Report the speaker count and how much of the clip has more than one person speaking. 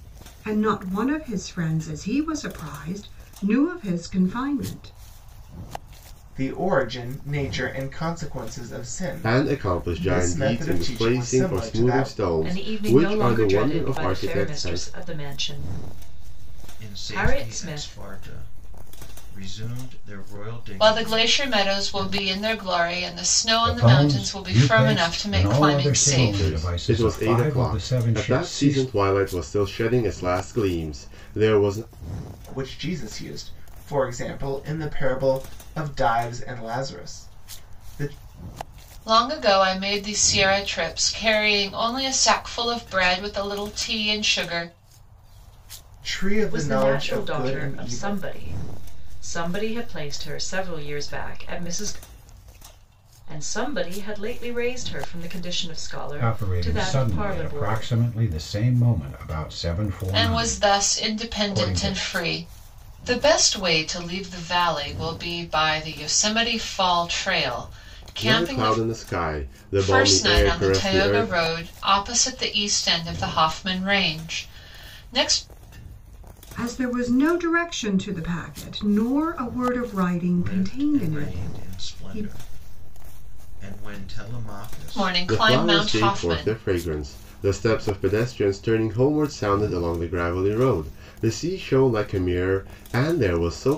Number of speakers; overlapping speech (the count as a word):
seven, about 26%